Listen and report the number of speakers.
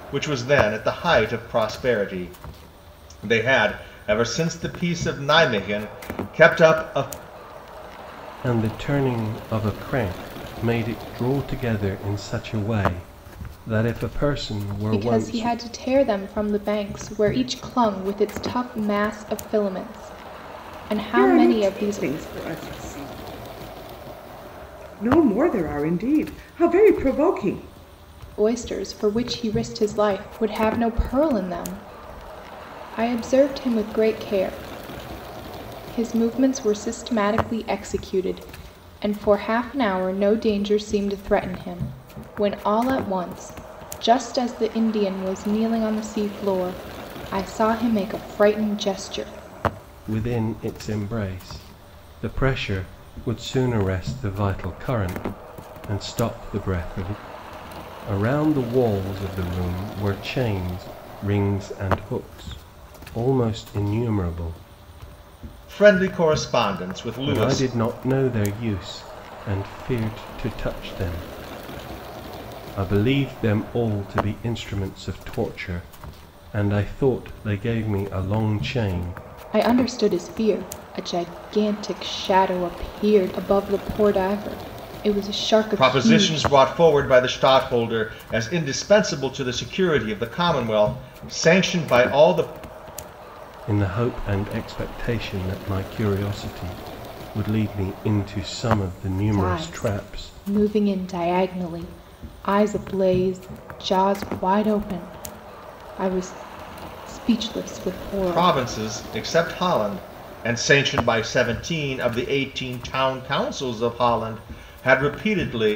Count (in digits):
4